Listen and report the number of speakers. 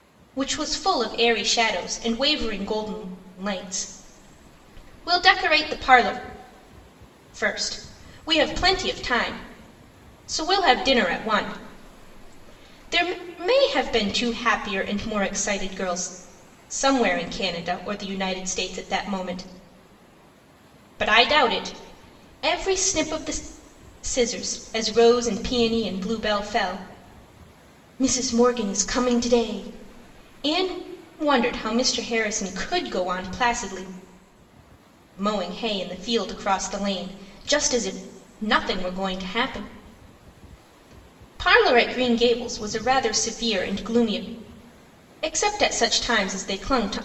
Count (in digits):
1